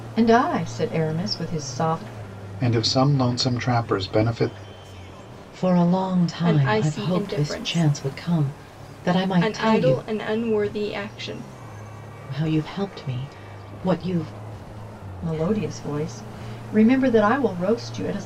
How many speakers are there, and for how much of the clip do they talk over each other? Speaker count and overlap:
4, about 12%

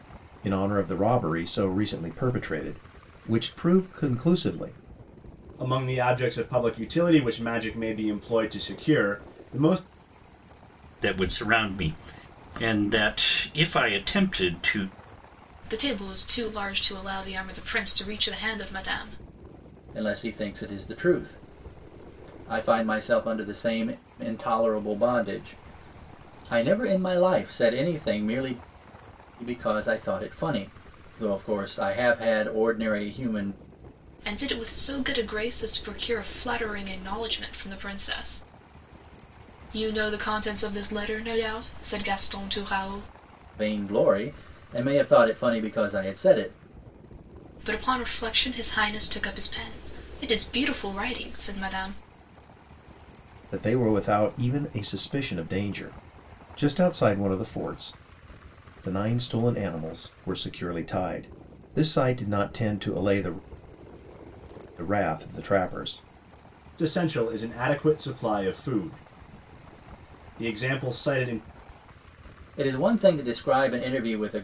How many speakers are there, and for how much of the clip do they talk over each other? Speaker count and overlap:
5, no overlap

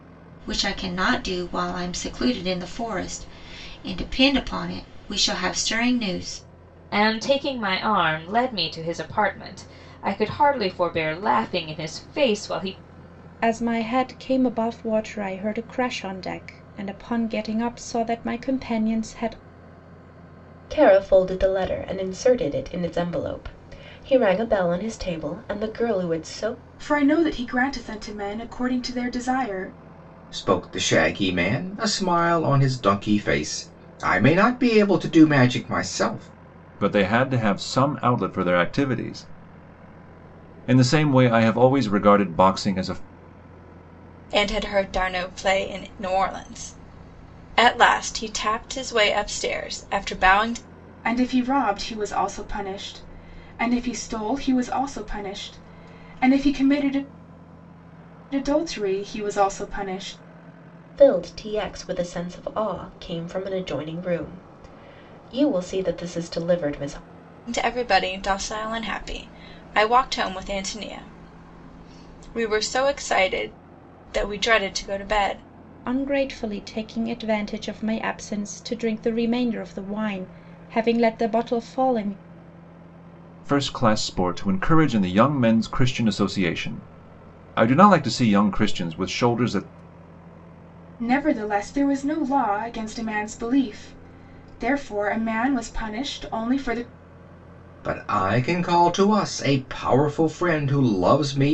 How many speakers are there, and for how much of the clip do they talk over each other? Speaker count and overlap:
8, no overlap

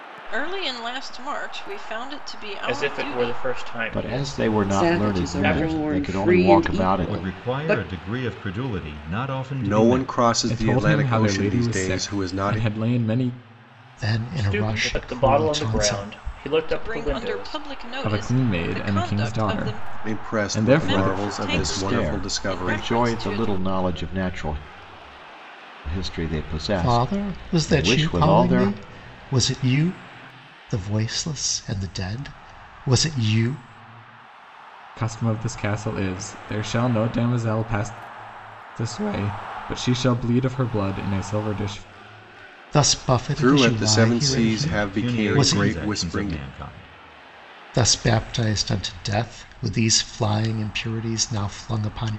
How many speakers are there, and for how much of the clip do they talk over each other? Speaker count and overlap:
8, about 40%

